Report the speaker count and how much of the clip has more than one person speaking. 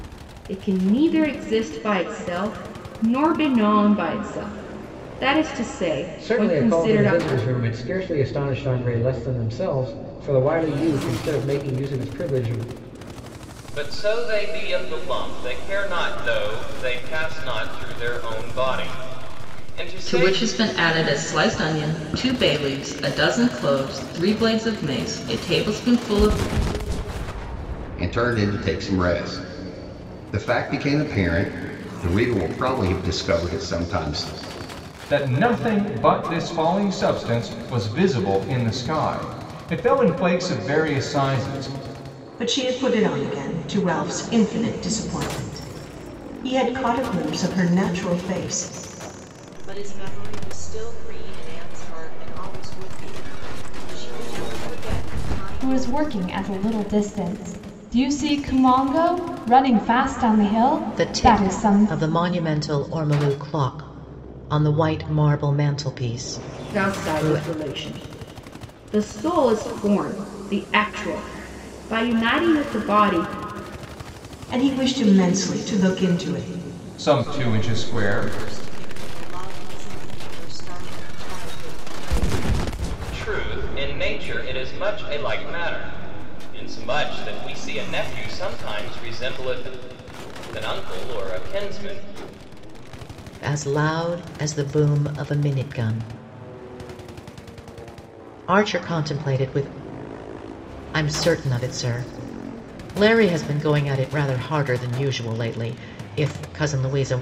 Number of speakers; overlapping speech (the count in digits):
10, about 4%